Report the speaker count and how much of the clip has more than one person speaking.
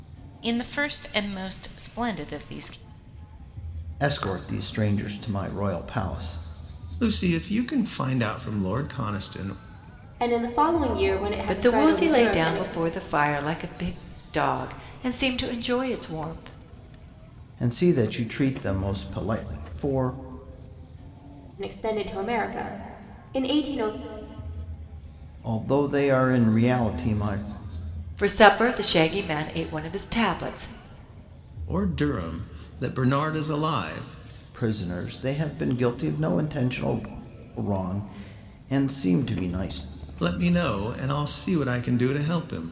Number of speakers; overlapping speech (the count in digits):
5, about 3%